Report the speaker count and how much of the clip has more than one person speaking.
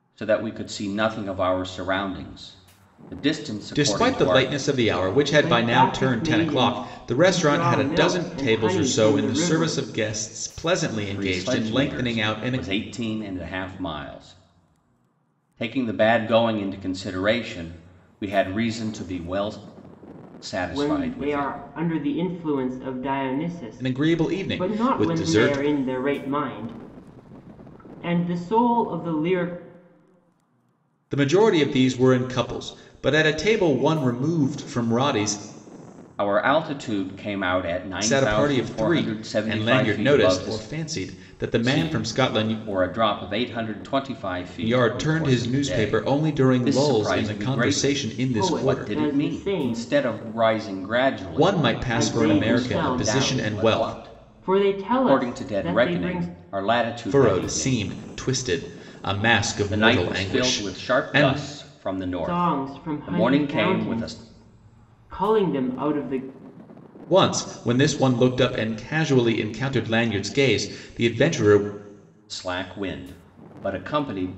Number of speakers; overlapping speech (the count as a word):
three, about 37%